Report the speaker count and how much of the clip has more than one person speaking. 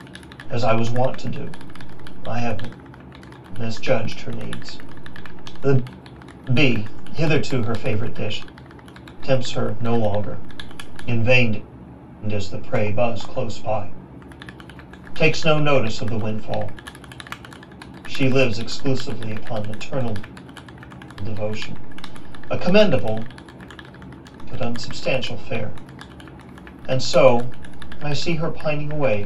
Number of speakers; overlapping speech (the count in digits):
1, no overlap